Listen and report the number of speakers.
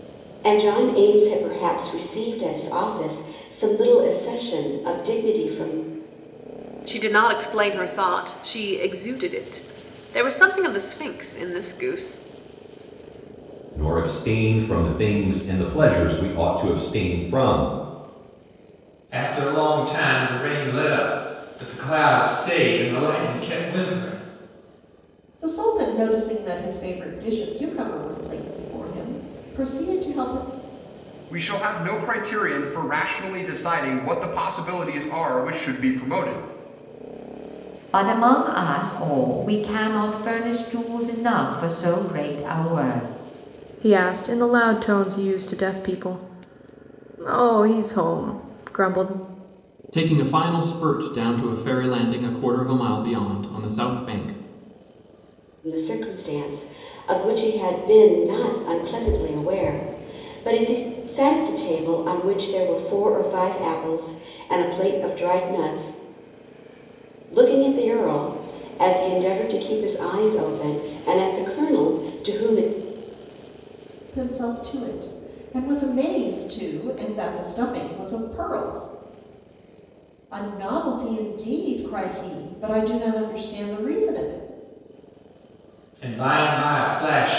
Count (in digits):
9